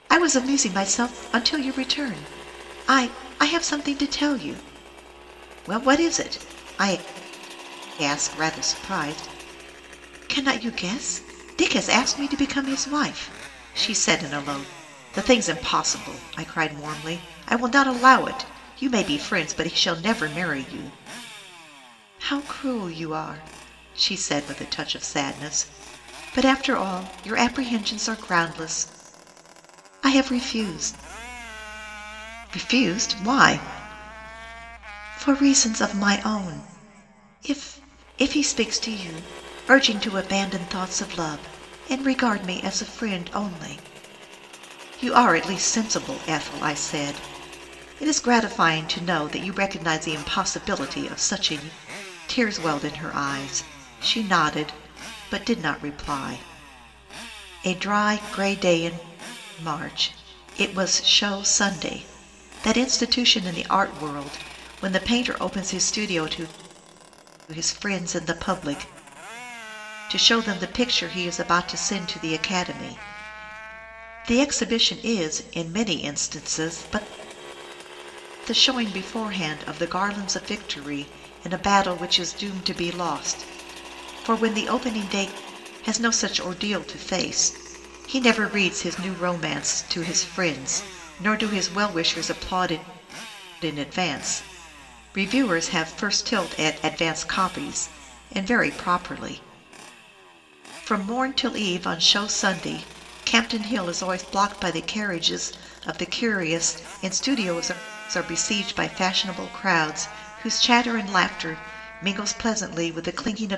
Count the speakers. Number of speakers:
one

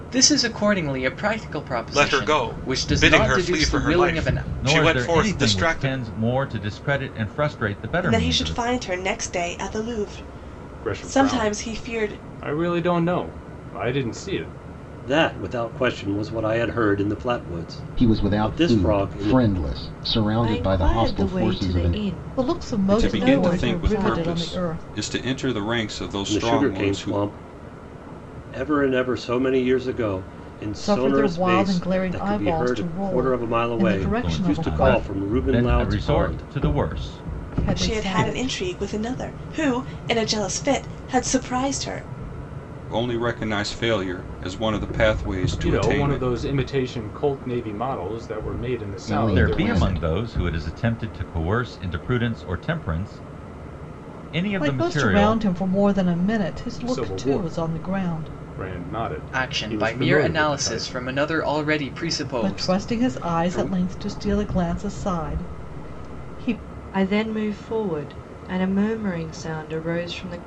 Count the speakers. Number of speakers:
ten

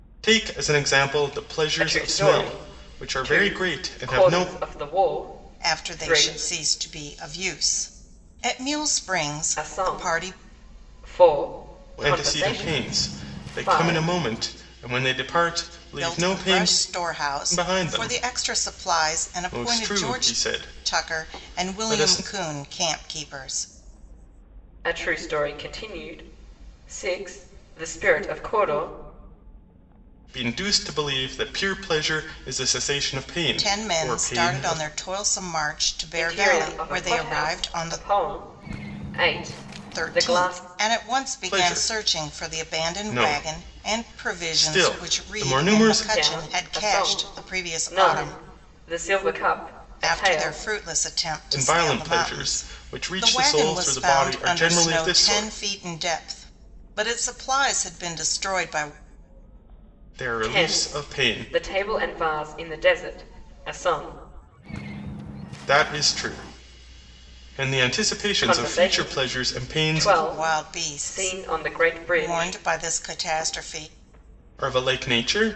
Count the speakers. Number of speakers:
three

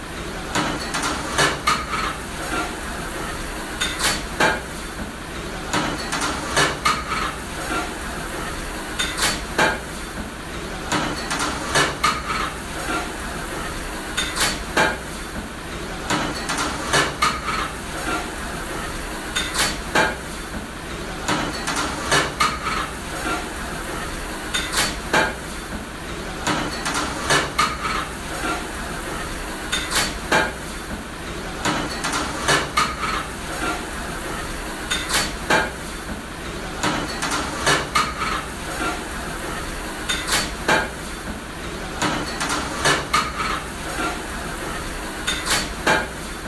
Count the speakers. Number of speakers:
zero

